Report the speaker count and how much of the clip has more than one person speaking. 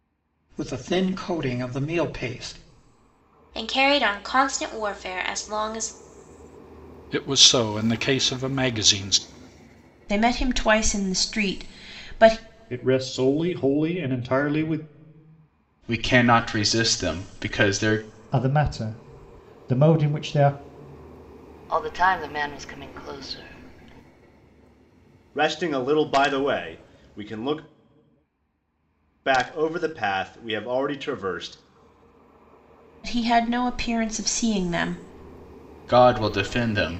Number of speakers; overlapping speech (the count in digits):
9, no overlap